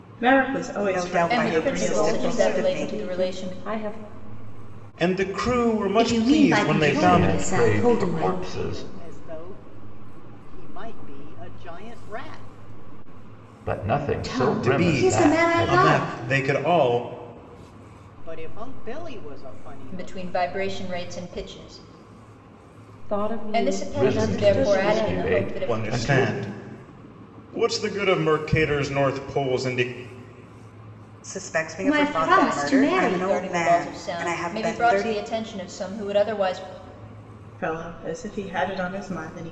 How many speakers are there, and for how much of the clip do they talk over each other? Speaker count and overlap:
8, about 37%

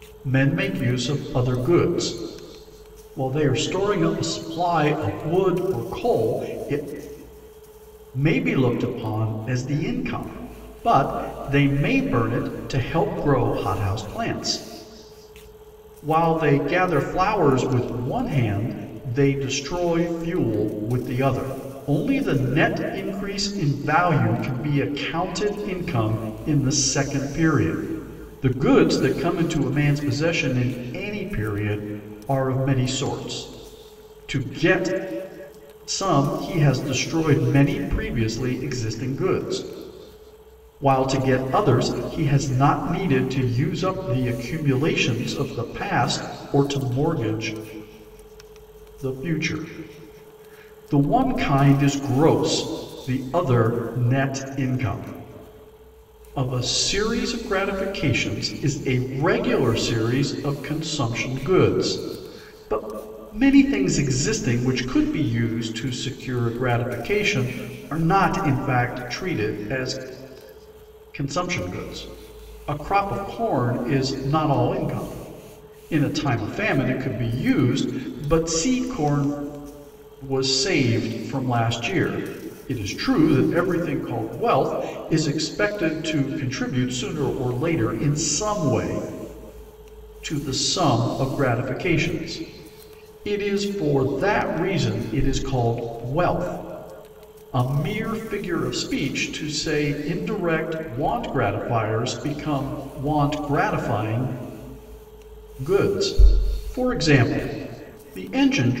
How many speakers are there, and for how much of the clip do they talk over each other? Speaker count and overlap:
1, no overlap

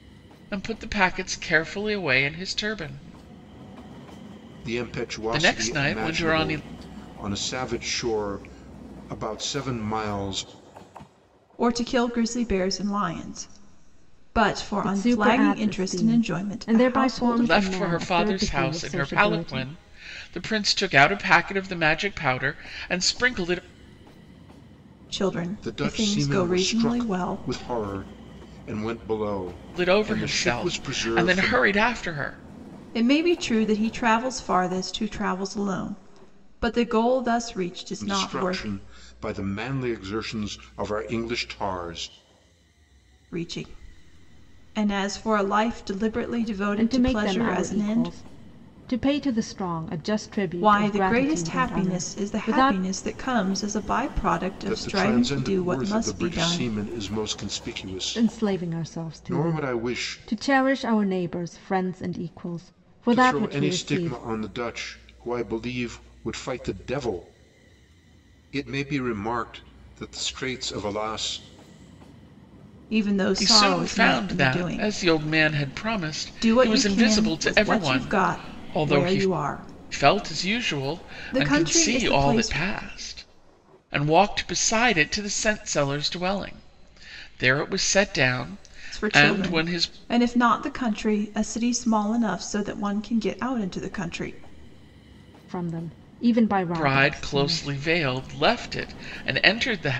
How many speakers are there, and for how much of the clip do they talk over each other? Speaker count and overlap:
4, about 30%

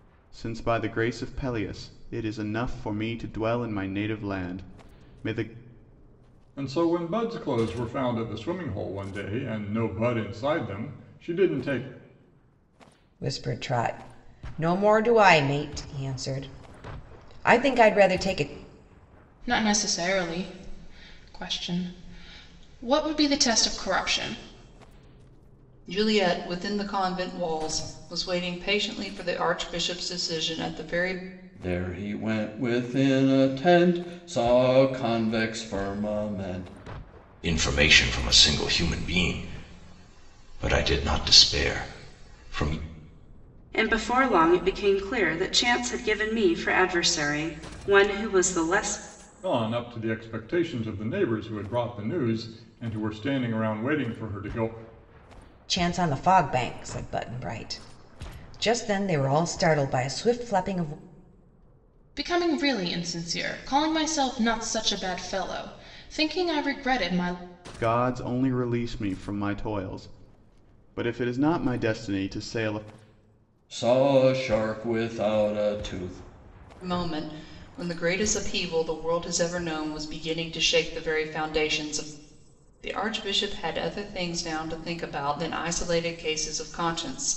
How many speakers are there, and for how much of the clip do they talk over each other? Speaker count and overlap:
8, no overlap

